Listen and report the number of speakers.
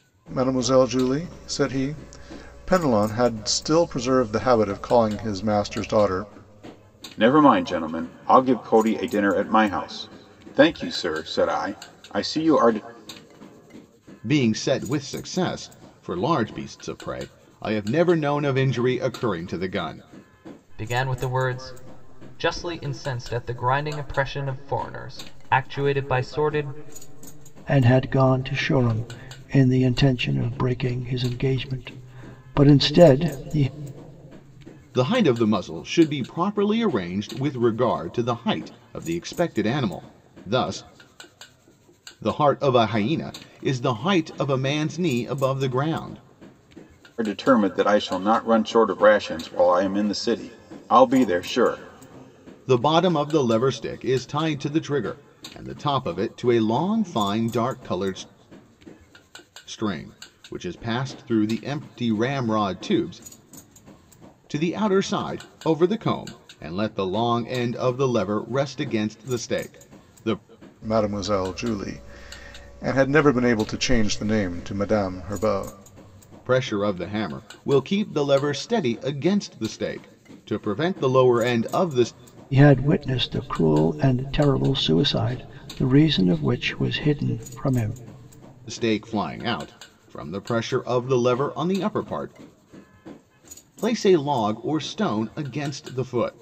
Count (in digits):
5